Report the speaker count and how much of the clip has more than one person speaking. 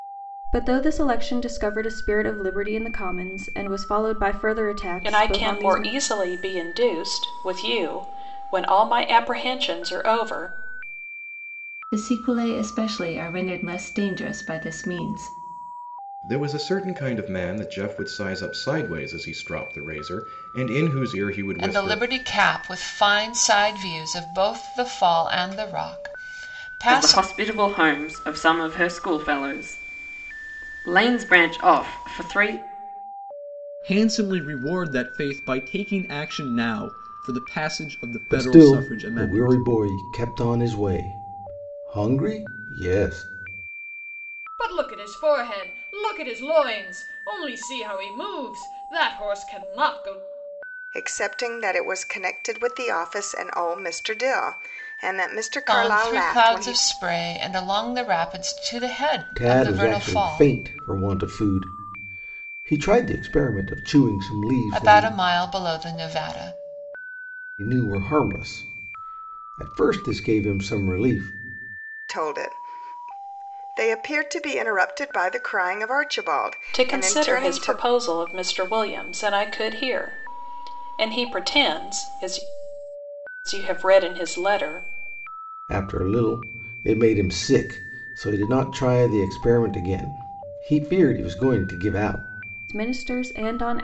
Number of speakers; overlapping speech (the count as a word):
ten, about 7%